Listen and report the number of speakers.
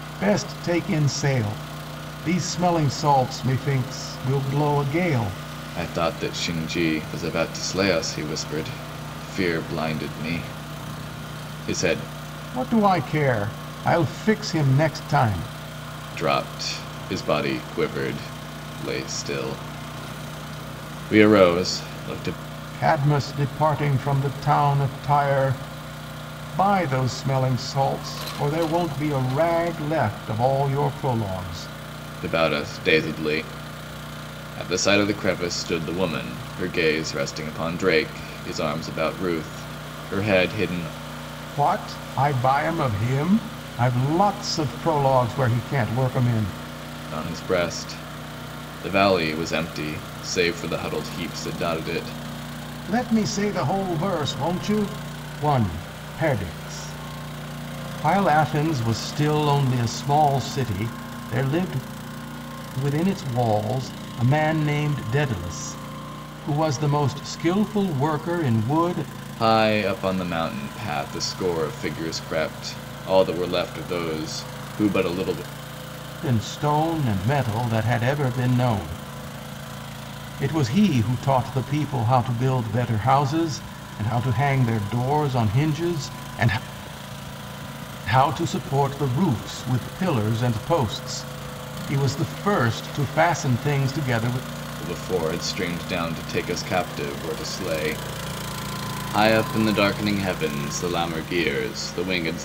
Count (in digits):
2